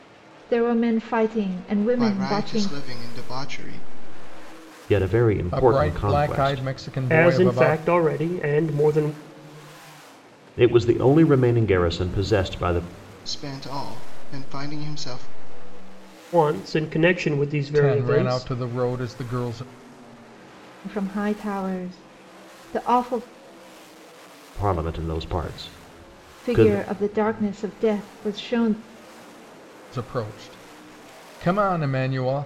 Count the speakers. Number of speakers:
5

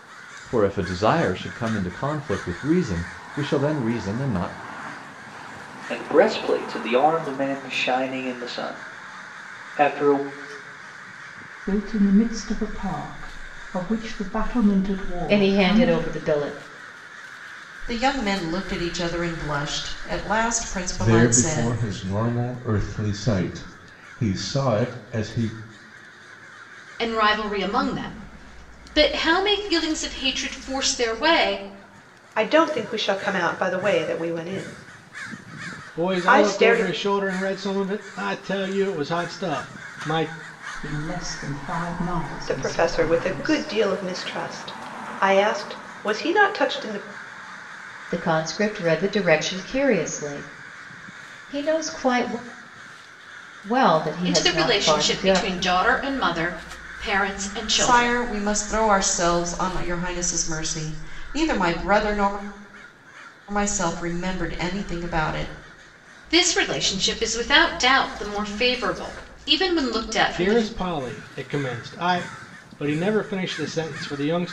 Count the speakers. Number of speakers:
9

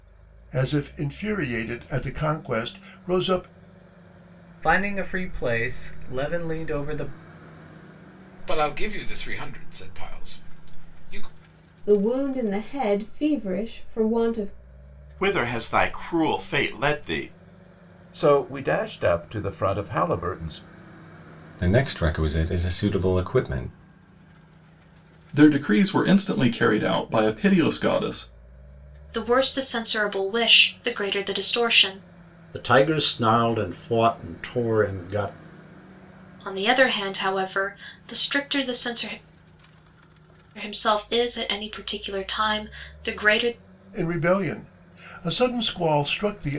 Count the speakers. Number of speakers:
10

